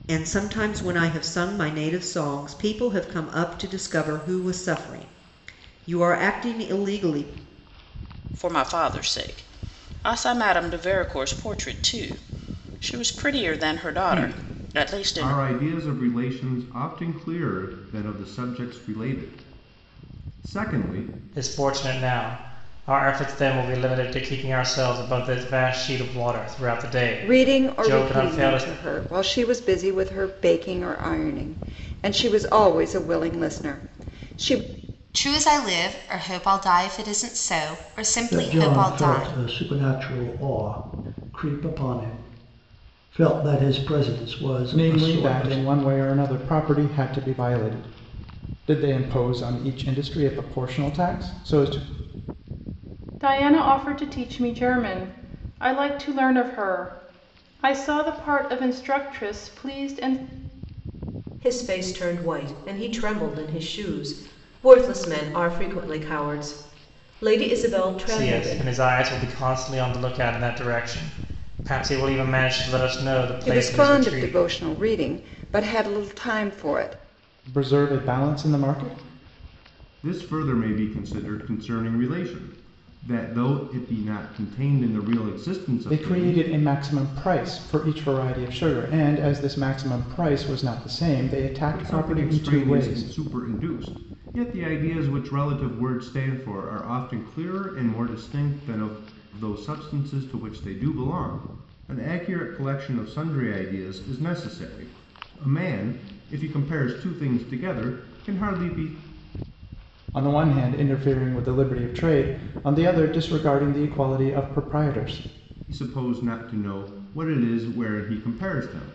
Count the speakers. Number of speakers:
ten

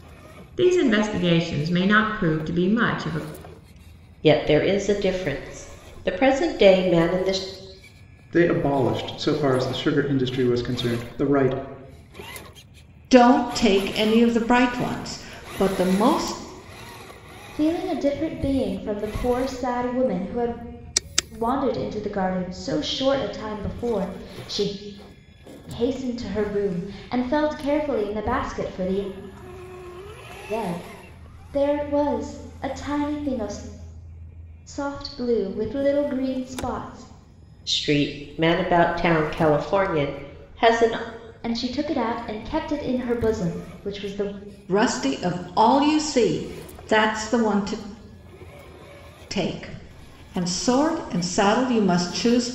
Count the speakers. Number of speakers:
five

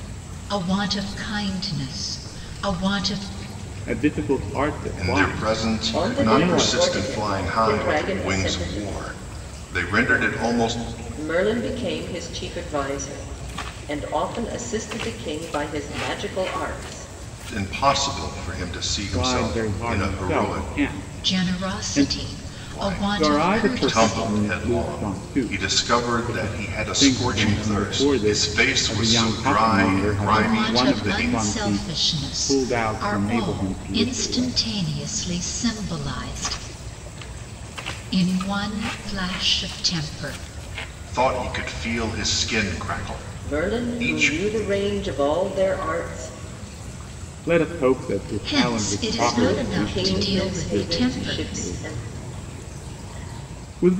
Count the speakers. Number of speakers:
four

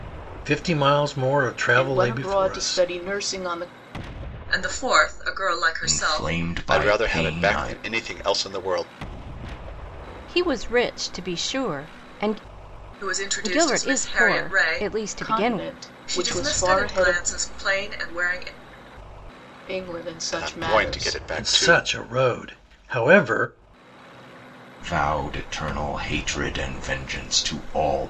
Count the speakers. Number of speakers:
six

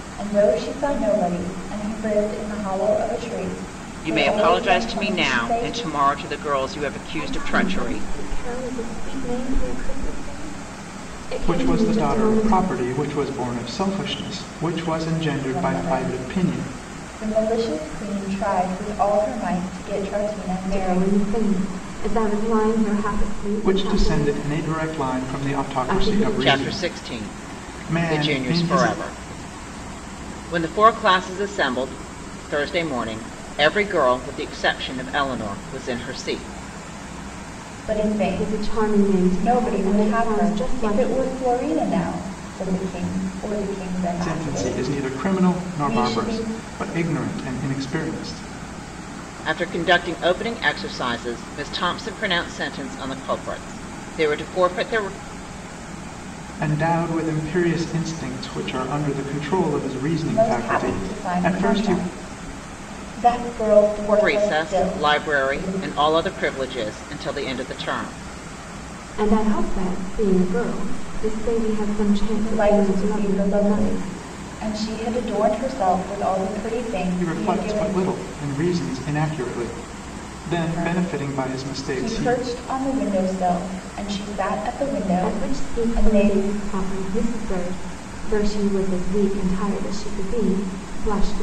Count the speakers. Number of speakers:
four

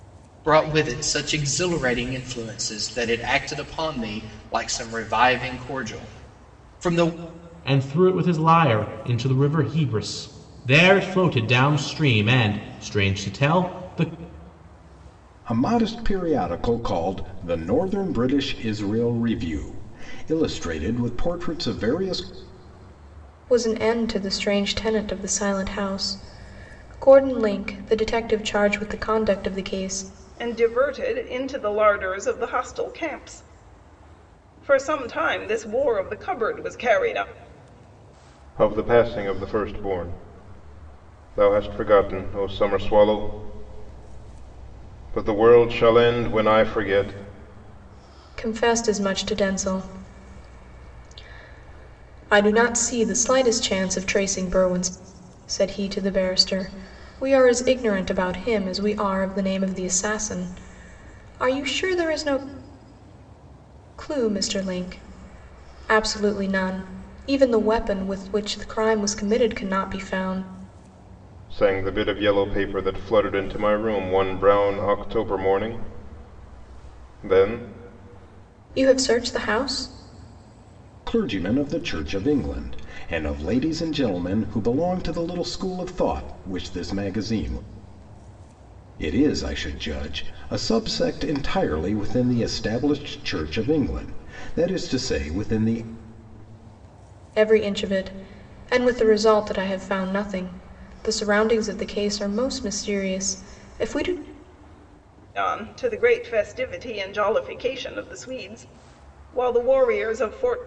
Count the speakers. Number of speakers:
six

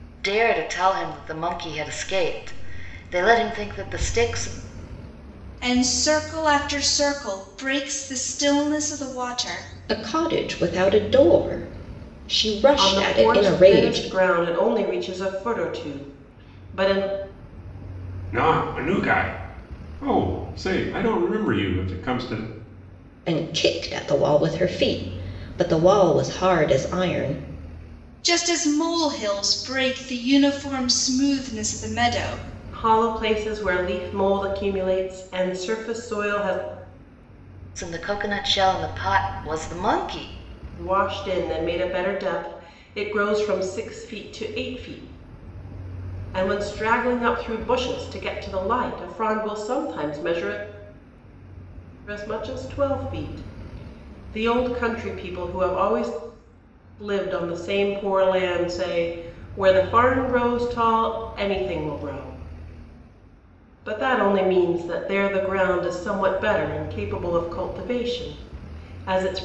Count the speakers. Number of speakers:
five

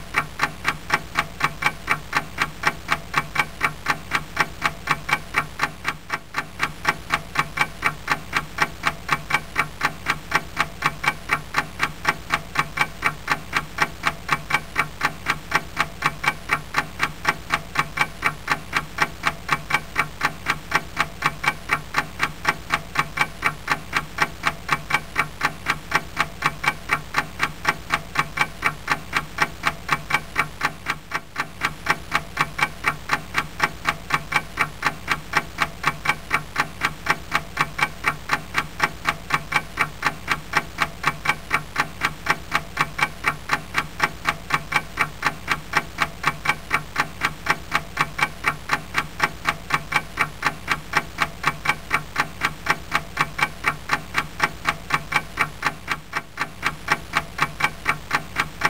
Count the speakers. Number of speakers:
zero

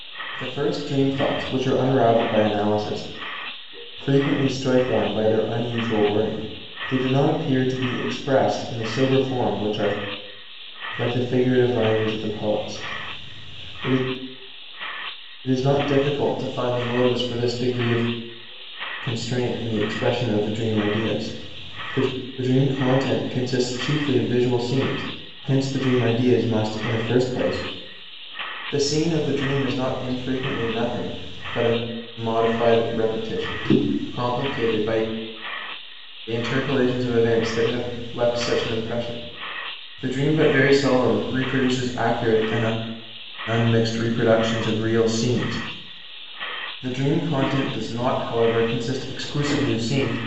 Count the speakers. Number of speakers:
one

